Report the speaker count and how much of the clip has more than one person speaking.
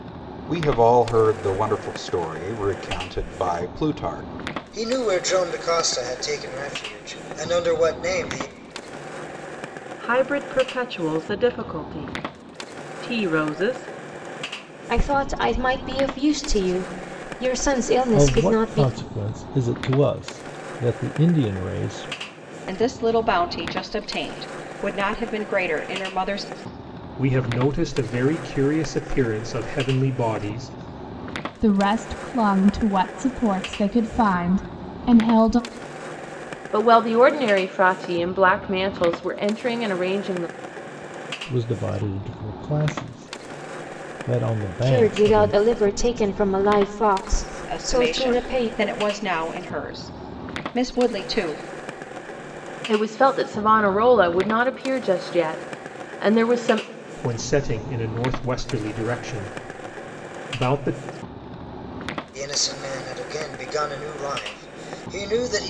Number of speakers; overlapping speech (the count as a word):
nine, about 4%